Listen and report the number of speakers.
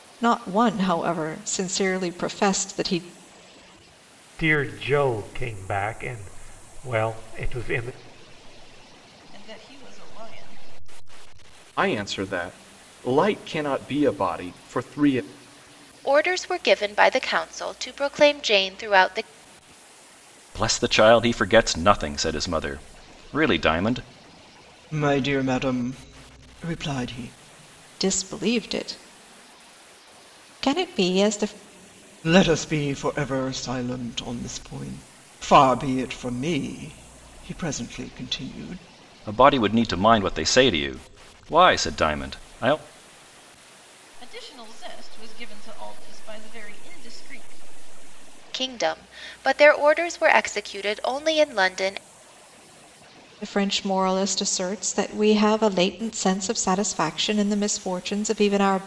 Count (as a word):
seven